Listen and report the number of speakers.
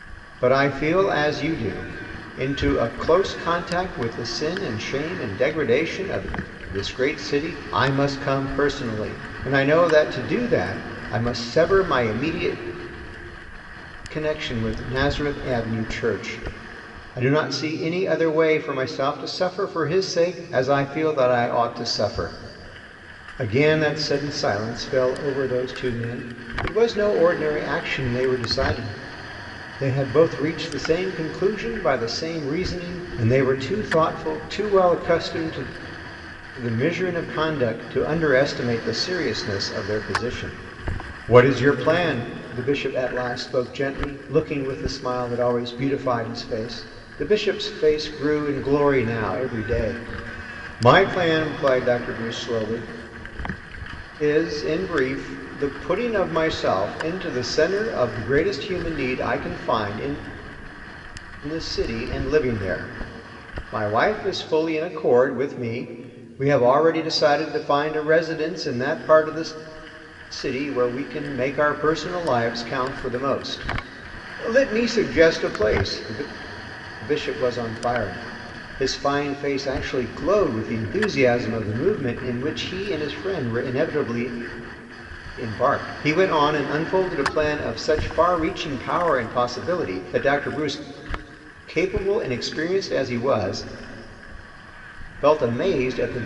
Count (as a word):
one